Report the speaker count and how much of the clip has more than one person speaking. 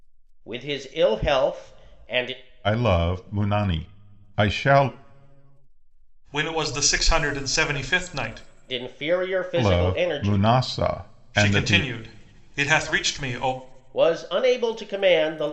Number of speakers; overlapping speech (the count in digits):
3, about 9%